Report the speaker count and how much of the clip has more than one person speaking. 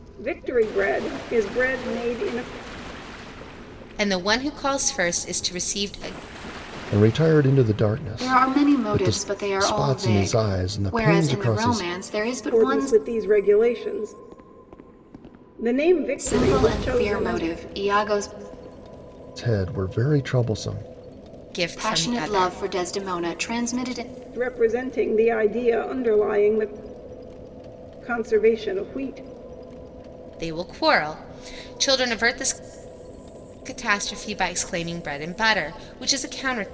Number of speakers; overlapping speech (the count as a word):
four, about 16%